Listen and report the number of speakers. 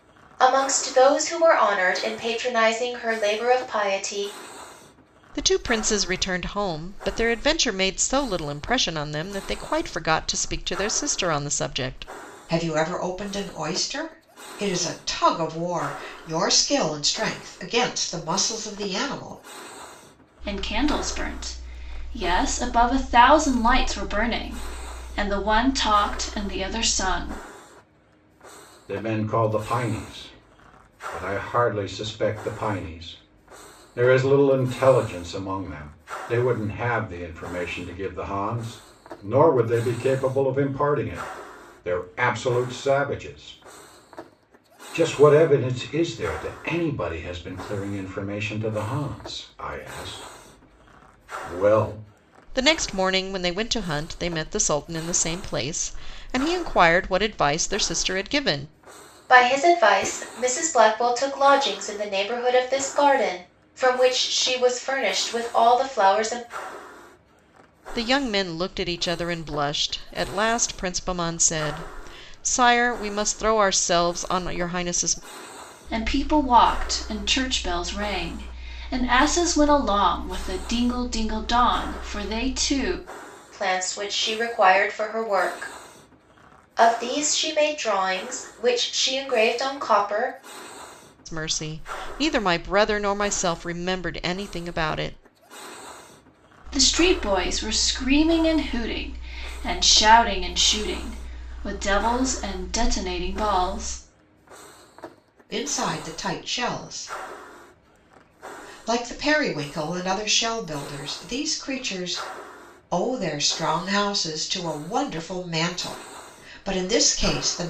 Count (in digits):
5